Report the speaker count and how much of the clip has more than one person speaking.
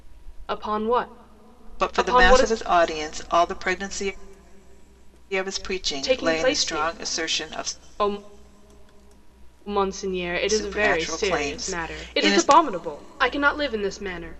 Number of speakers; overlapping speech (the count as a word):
two, about 33%